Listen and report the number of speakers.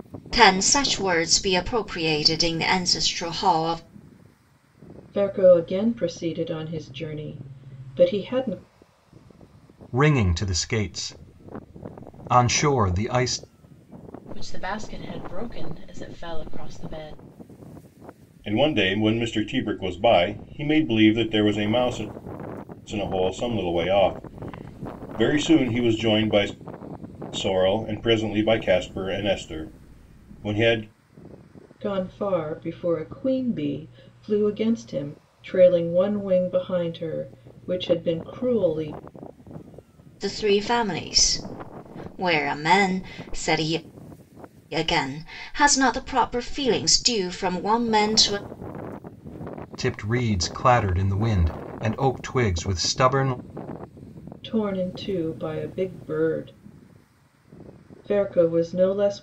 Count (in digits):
5